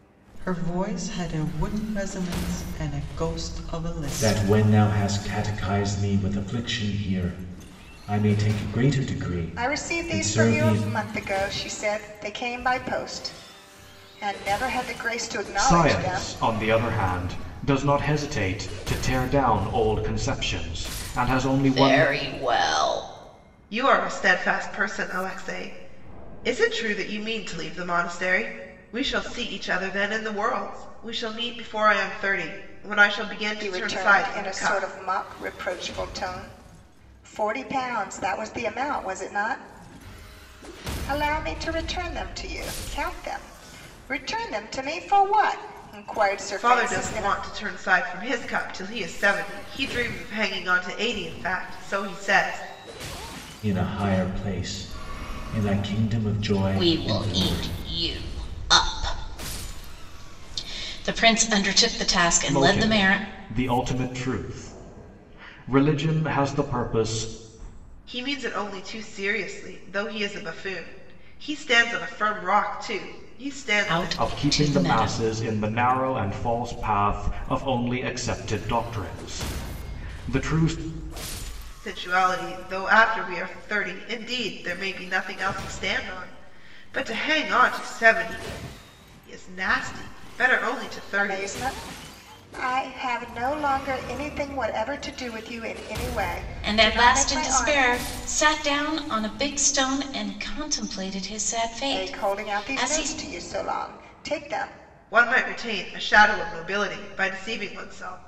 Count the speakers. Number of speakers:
six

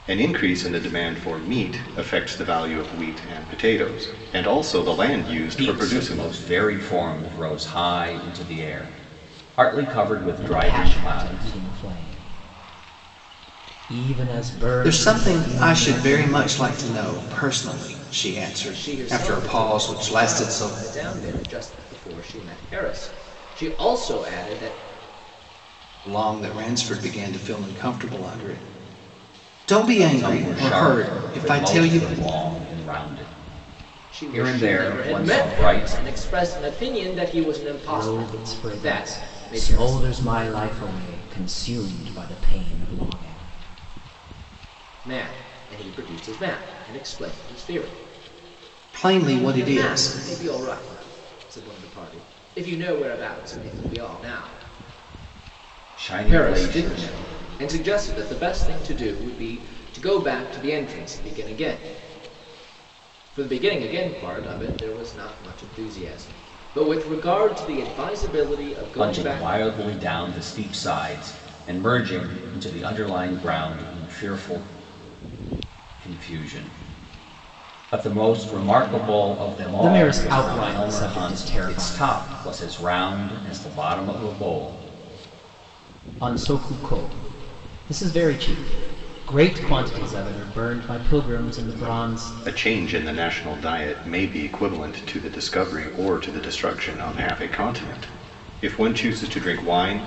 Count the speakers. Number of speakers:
five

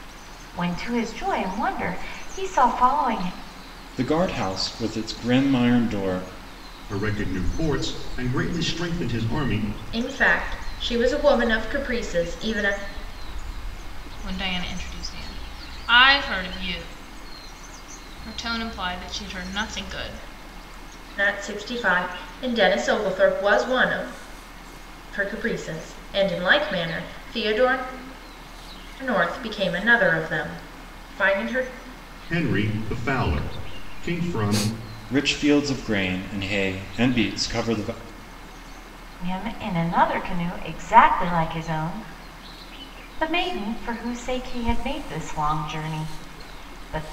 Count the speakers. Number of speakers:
five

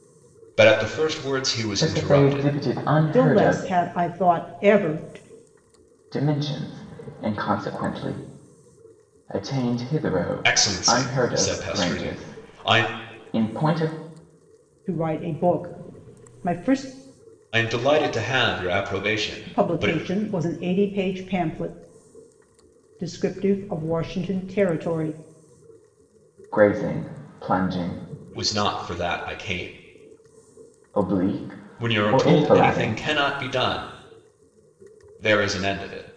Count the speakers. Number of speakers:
three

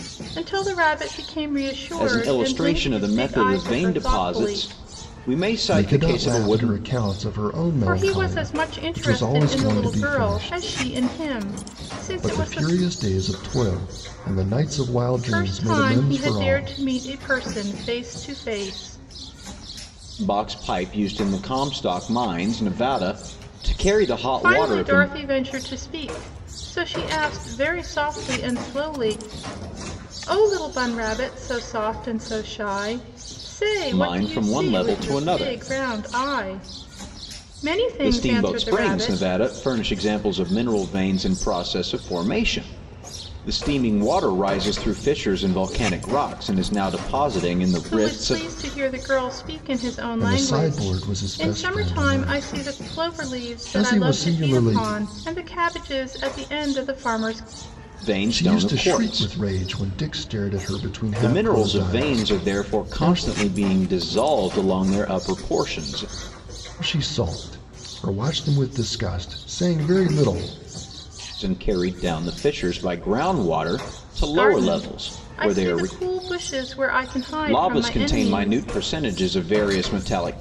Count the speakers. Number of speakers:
three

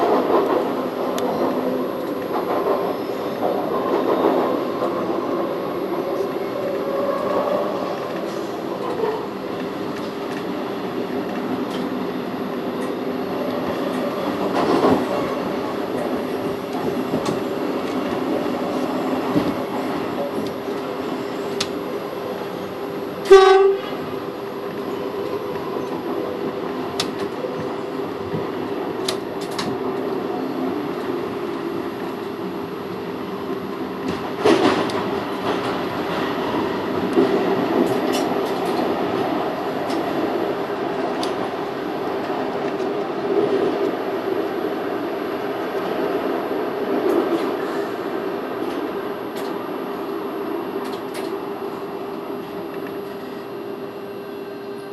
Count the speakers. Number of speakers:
zero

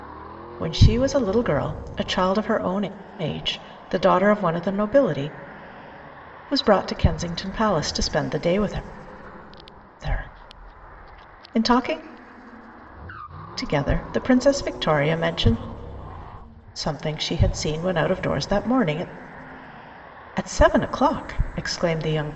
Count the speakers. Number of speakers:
one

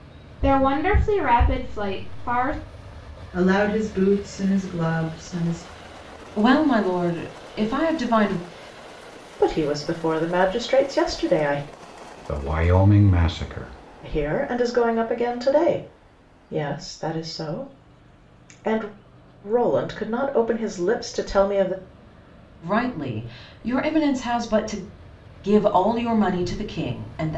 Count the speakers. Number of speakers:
five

